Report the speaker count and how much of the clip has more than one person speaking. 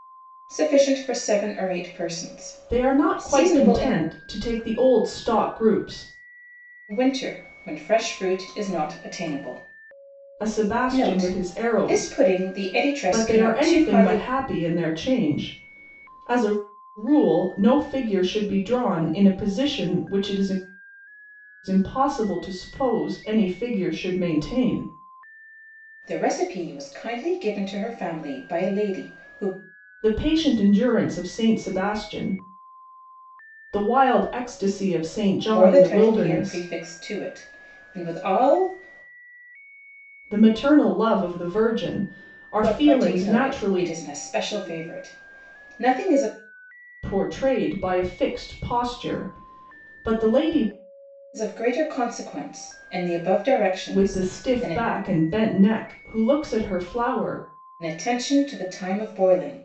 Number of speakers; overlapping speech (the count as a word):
two, about 12%